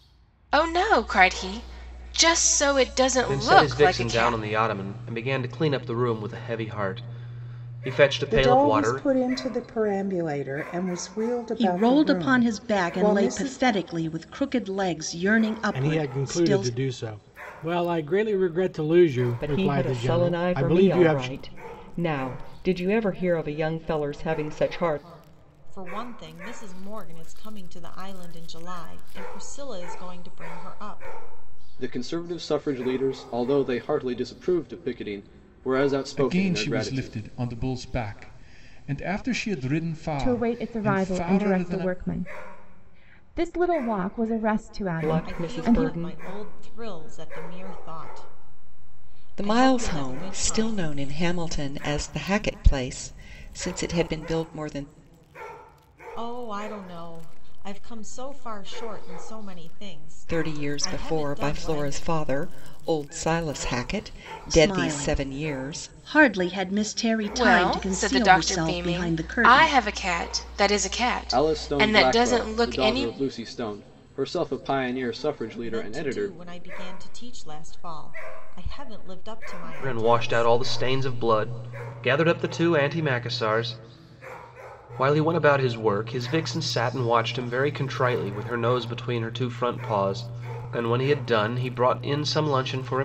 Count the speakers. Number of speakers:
10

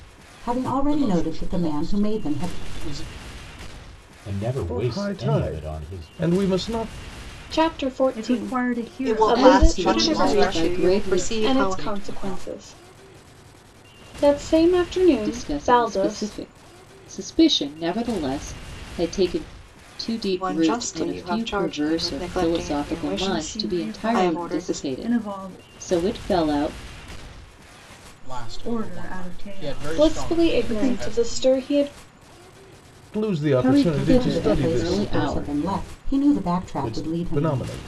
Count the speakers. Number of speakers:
9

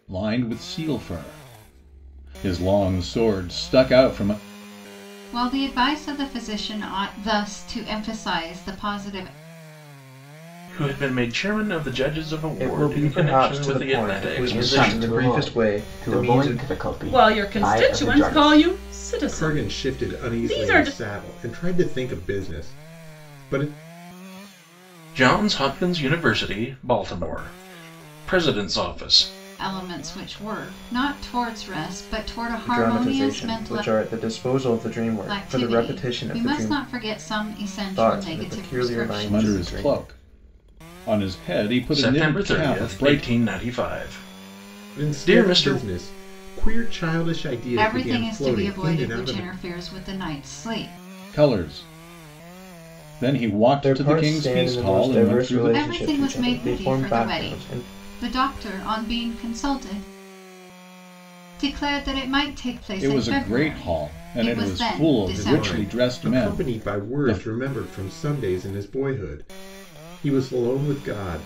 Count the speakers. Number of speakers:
7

